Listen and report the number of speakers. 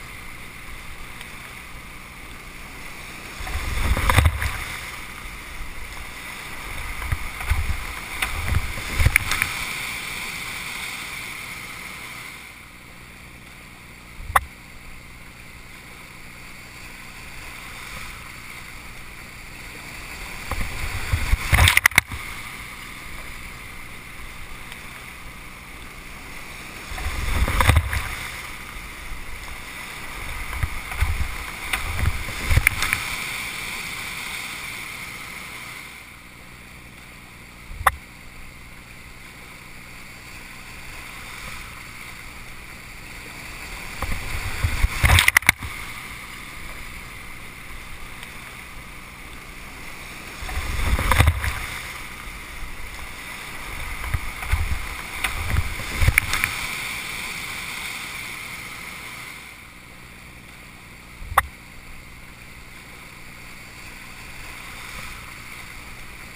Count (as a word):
zero